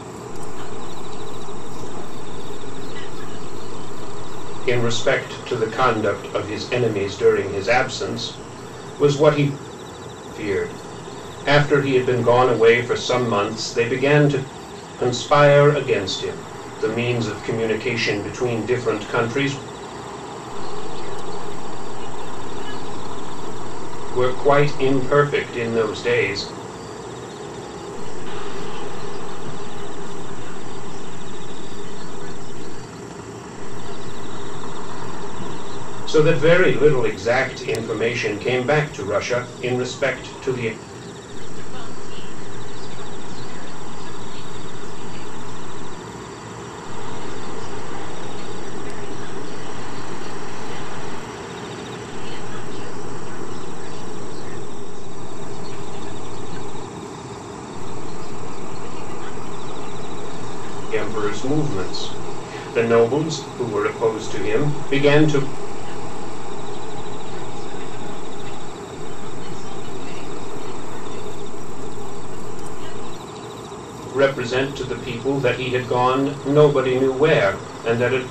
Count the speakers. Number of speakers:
2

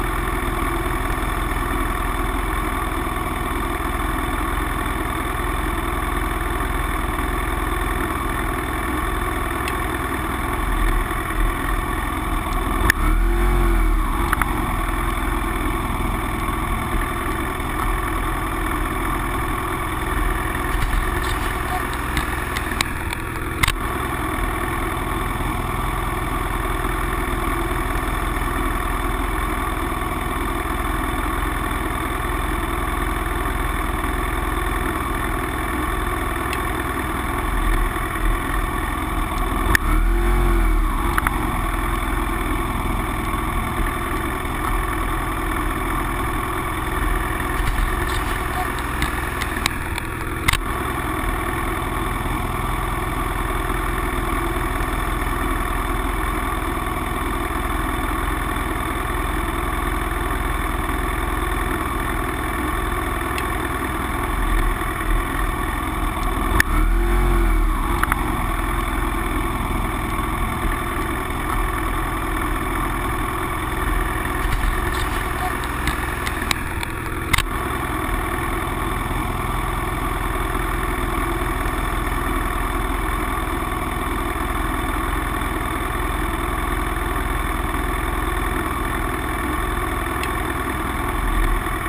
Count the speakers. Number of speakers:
0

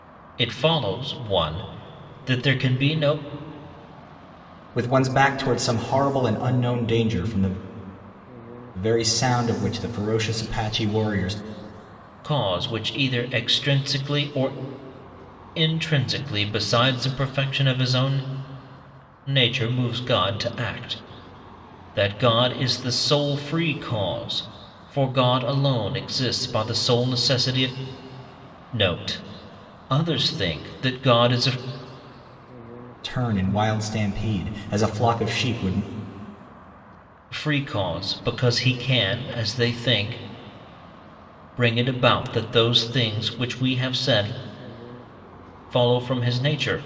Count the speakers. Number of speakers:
2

